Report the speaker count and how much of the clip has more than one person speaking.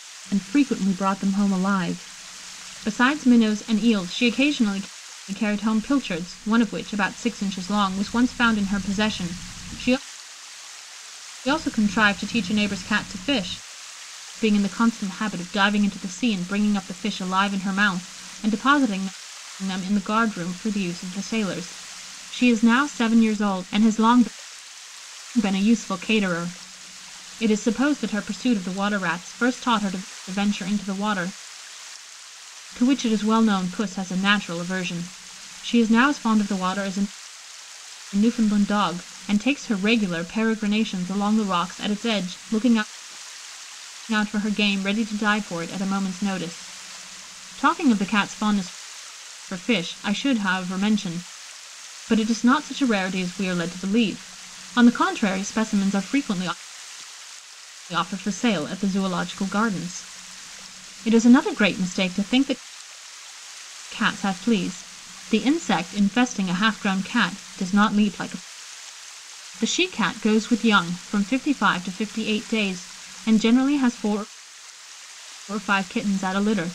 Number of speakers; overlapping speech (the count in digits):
1, no overlap